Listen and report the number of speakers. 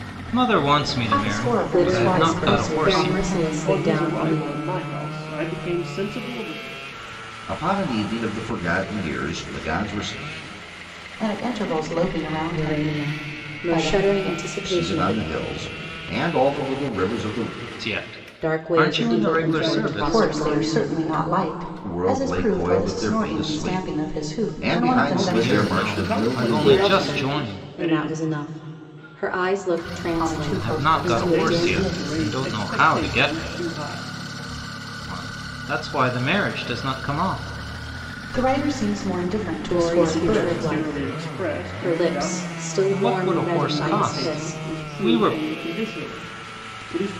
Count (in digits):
5